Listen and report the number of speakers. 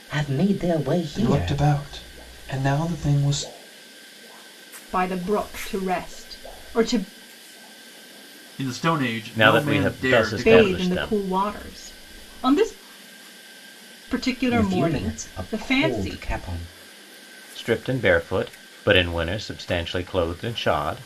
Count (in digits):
5